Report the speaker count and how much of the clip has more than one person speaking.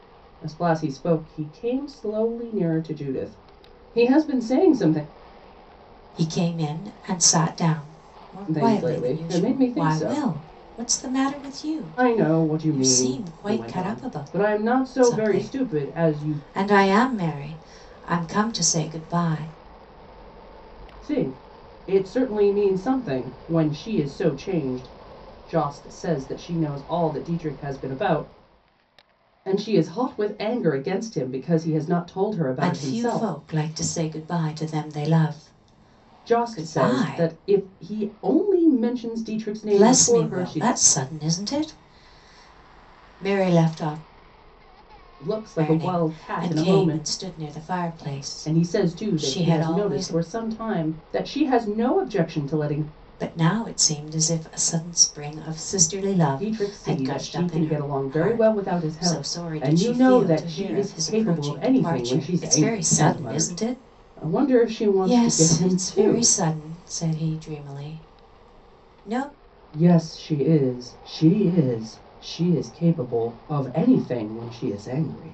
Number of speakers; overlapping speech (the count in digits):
2, about 27%